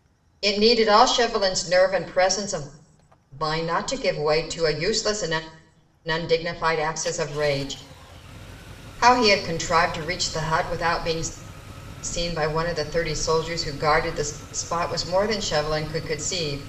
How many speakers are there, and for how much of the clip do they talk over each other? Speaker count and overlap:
one, no overlap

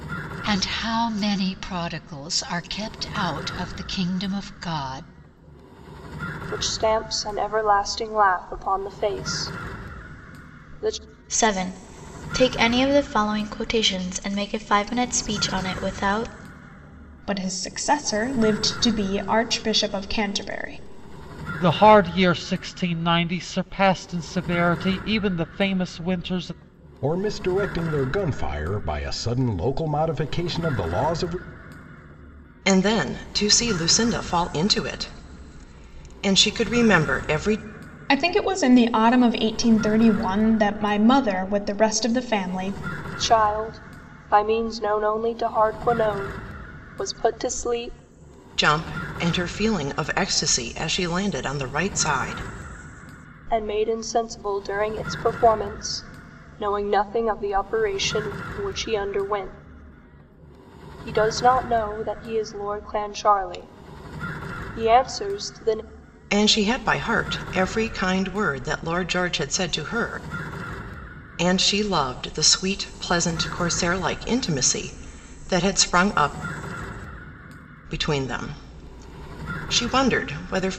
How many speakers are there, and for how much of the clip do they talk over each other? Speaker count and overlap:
seven, no overlap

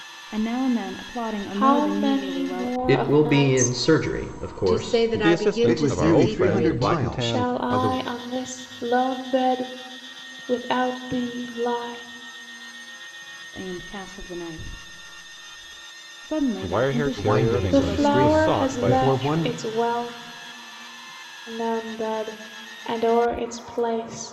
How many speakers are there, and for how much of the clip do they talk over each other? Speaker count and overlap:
six, about 35%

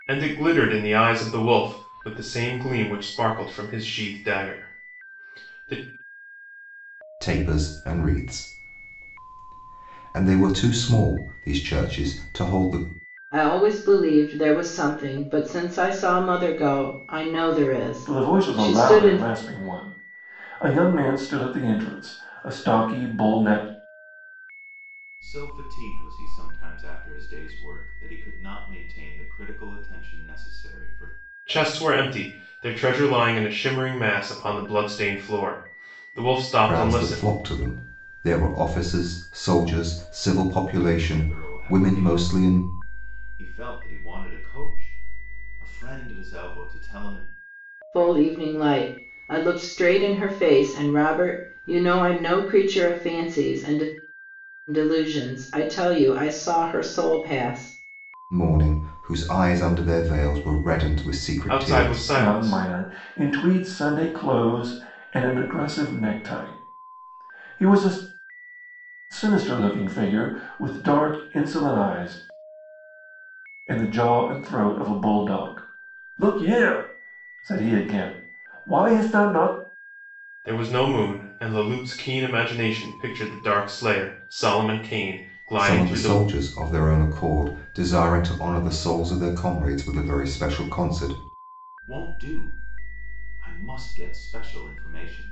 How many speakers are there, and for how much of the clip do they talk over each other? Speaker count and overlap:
five, about 6%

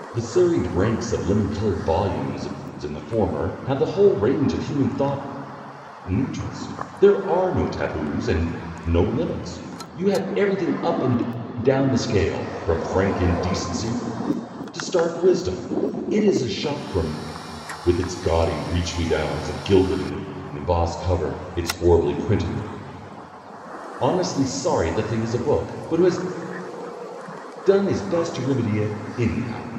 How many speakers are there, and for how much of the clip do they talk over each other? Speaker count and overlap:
one, no overlap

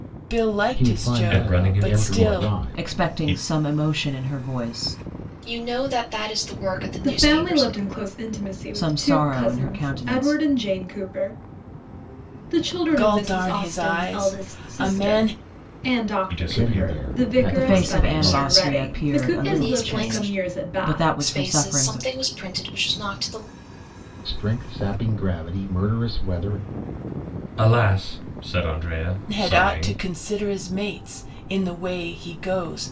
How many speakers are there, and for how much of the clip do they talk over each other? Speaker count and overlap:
six, about 43%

